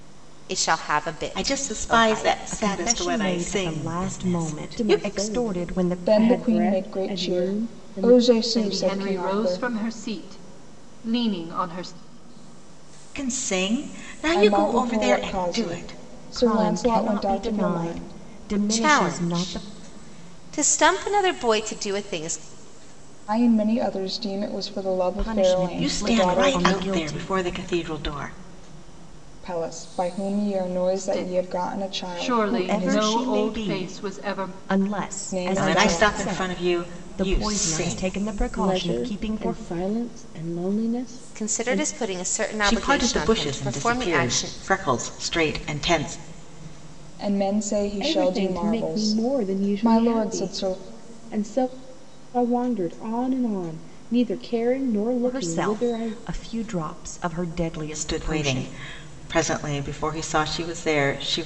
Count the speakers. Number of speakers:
six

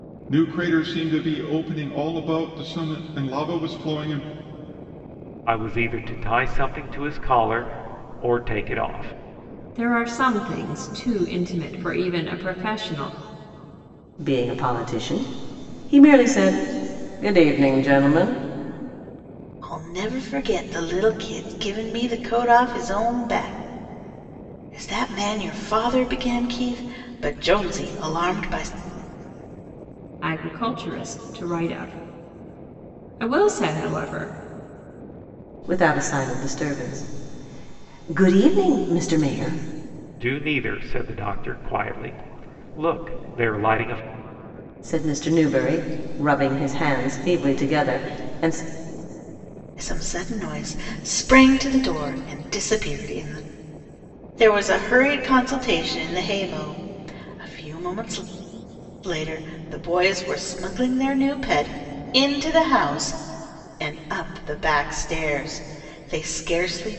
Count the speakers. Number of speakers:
five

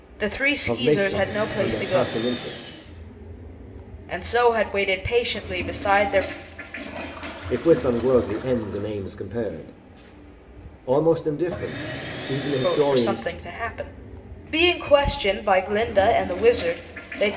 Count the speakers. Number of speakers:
two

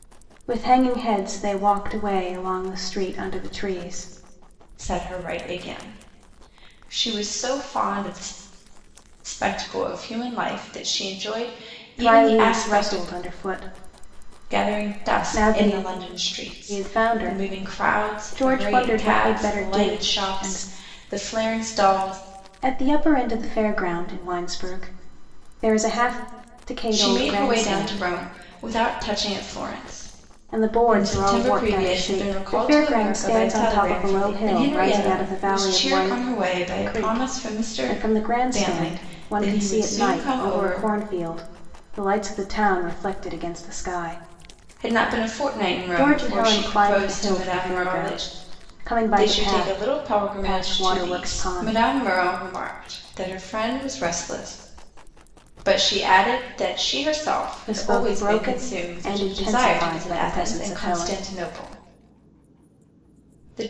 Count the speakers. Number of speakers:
two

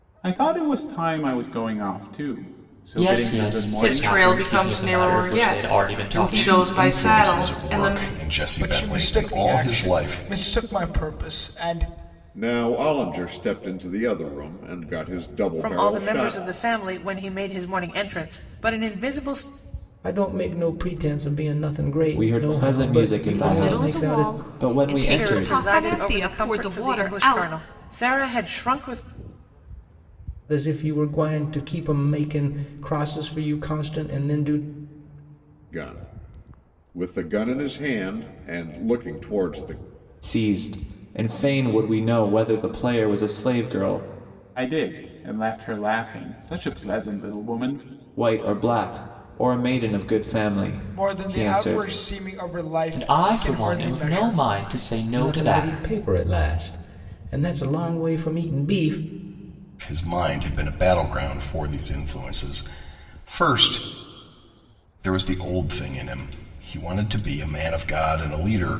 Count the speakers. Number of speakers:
ten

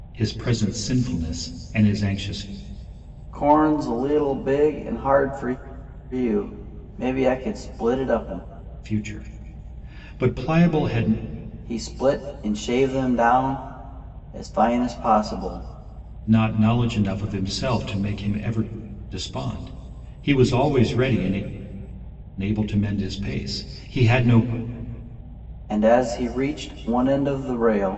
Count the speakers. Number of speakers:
two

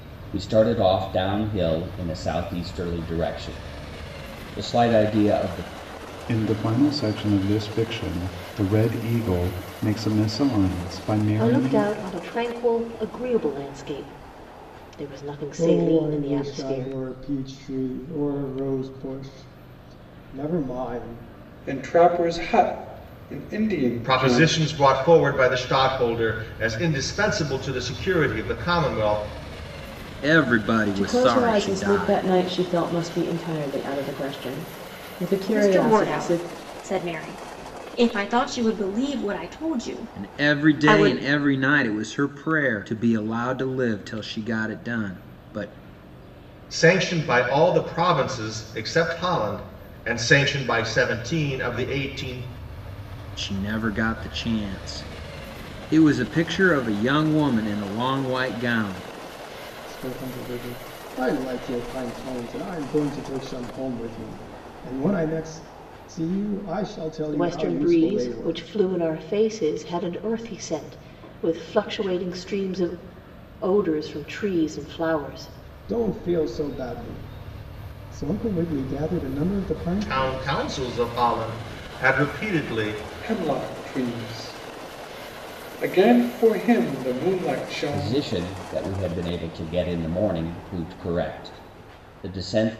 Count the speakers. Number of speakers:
nine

